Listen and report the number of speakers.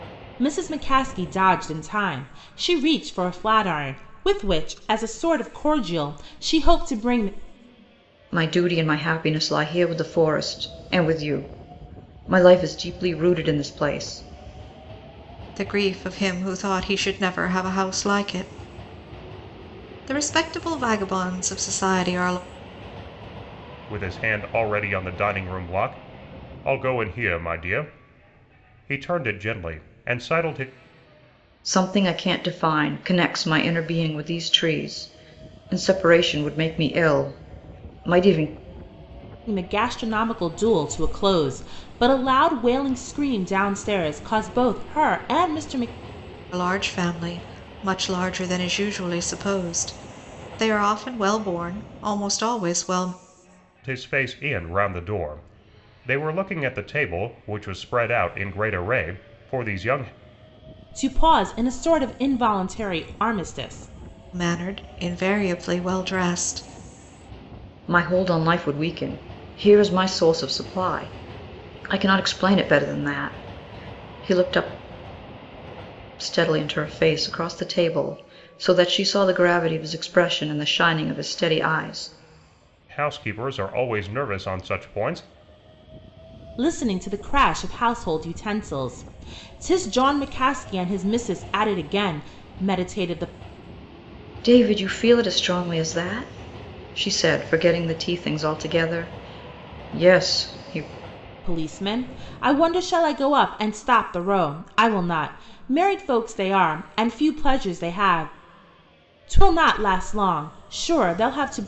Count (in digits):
4